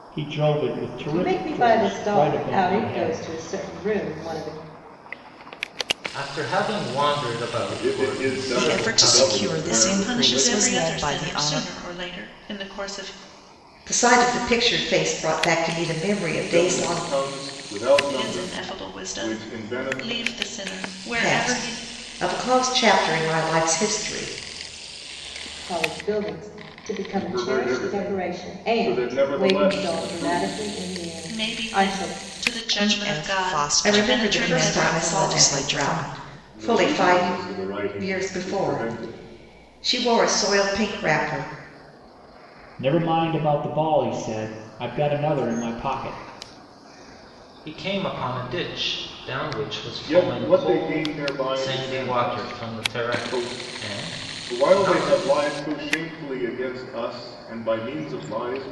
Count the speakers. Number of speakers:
seven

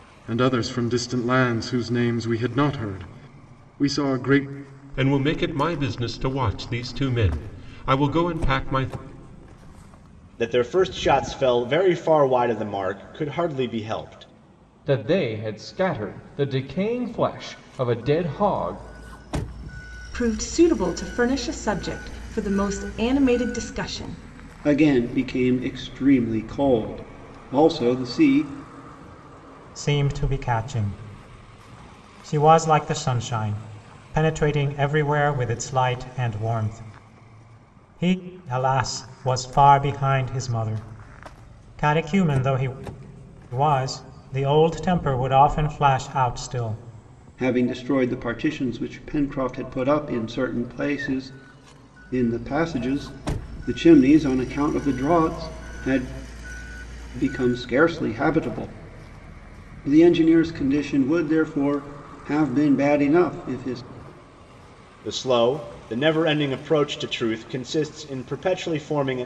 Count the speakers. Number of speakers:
seven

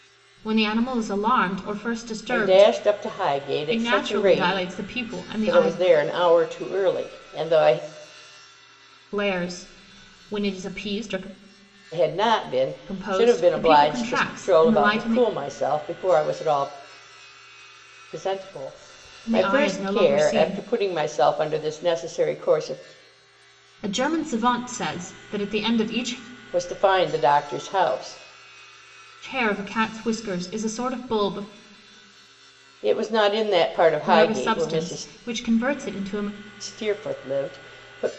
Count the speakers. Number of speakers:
two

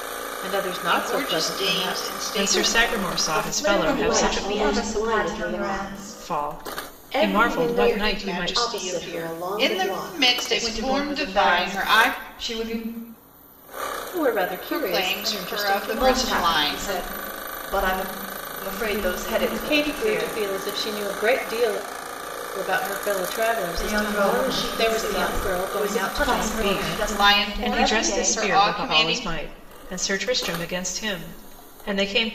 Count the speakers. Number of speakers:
five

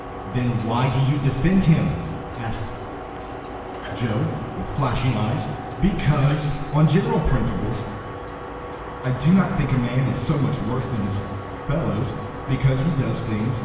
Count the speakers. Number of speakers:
one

